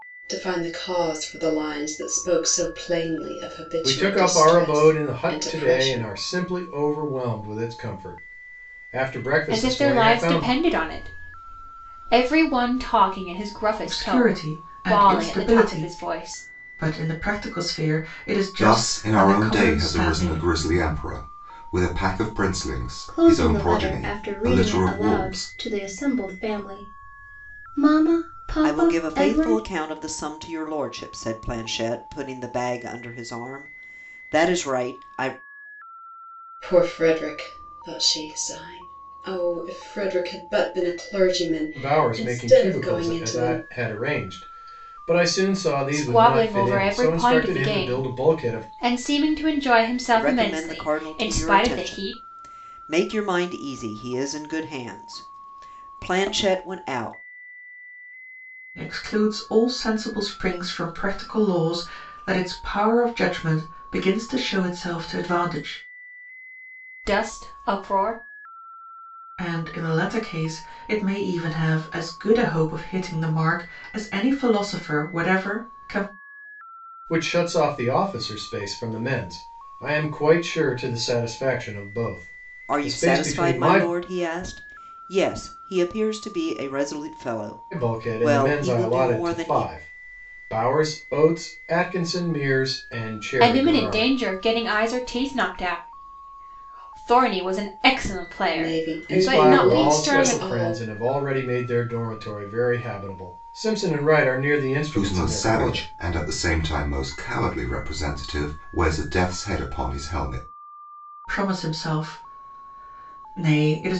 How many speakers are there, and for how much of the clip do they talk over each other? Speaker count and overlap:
7, about 22%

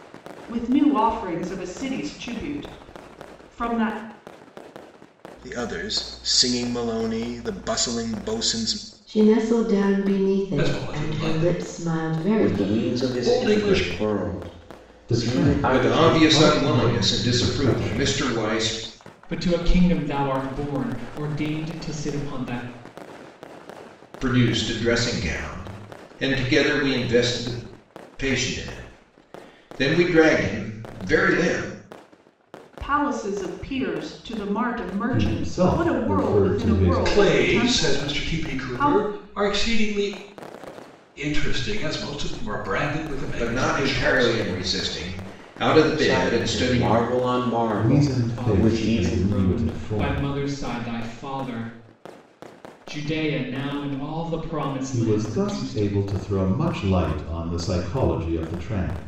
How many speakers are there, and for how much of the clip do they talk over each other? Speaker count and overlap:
8, about 27%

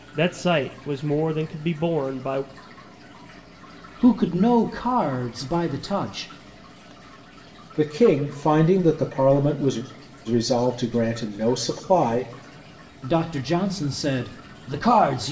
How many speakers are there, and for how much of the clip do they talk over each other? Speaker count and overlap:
3, no overlap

